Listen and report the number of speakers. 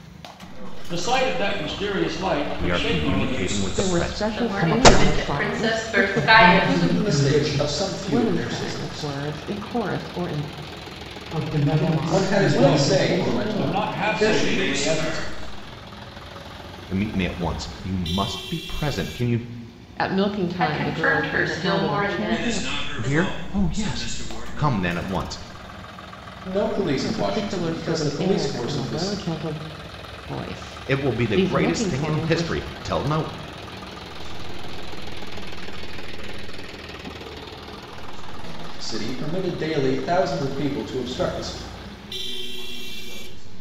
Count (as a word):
eight